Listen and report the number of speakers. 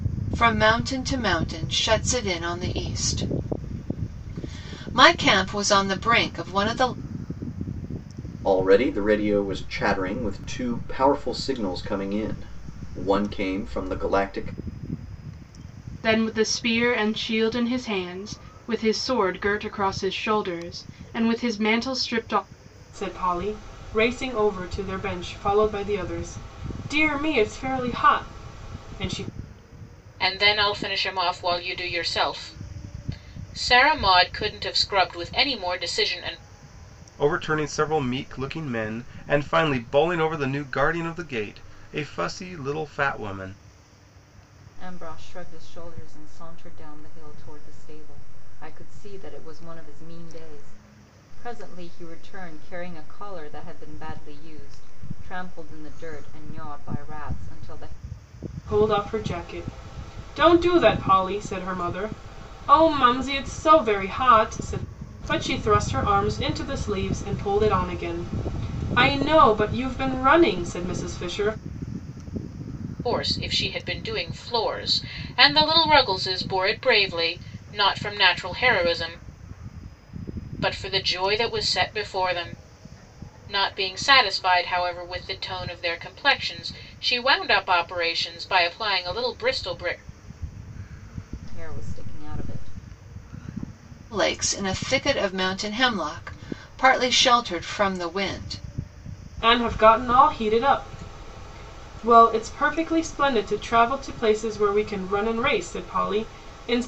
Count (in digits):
7